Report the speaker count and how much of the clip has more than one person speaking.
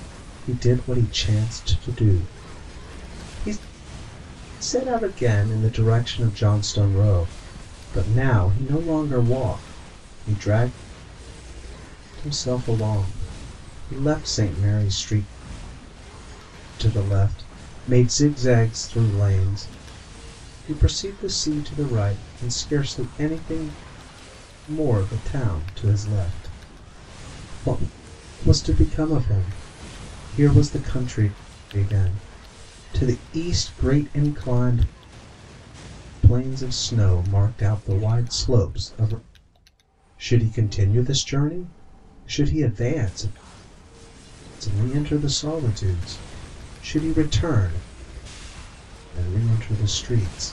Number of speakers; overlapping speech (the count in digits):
1, no overlap